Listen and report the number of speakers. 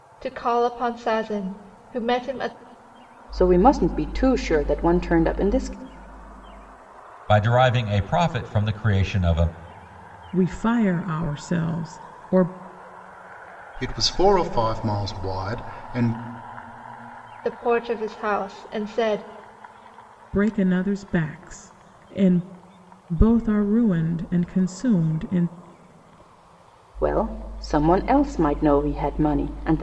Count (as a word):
five